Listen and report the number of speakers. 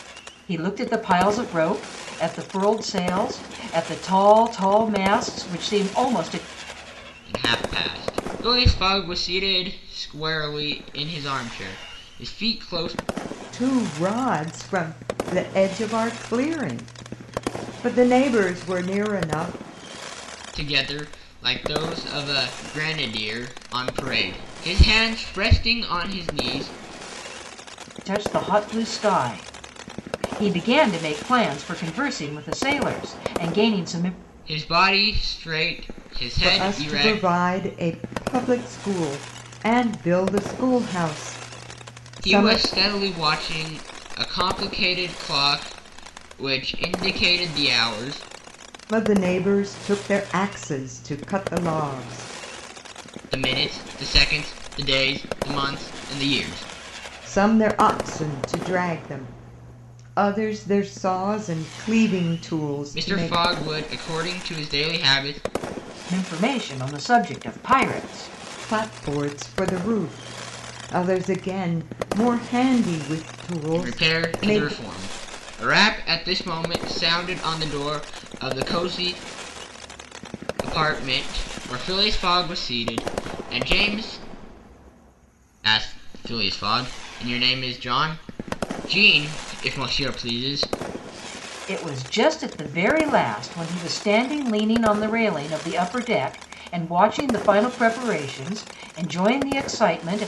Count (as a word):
three